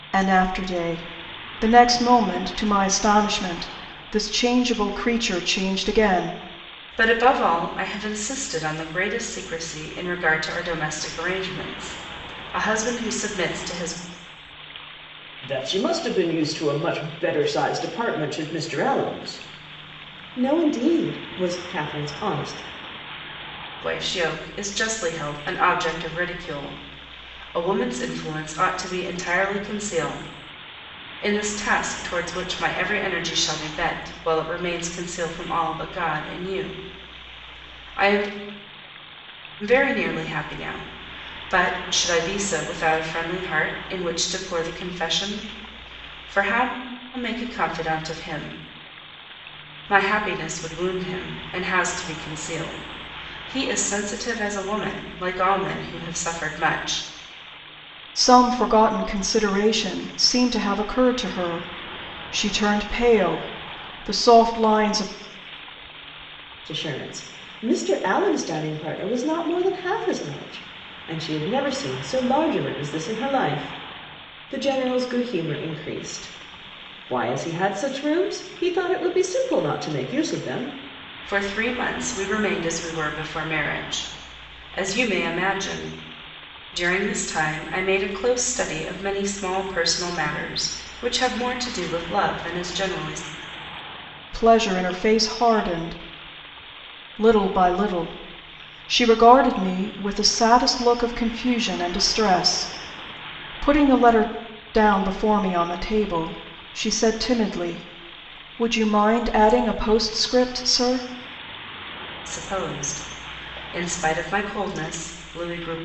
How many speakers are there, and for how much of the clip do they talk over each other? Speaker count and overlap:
3, no overlap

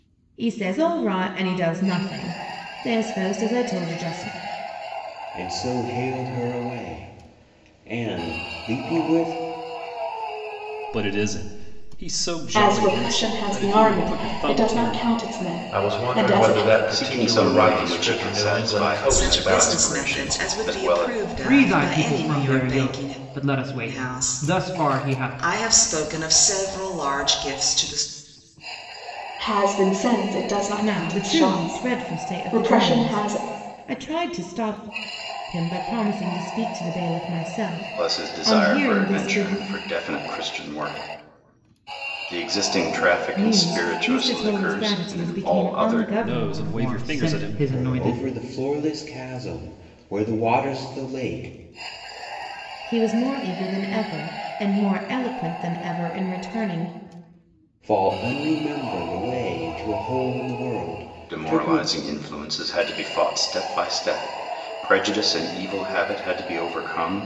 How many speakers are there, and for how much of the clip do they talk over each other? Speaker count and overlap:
8, about 31%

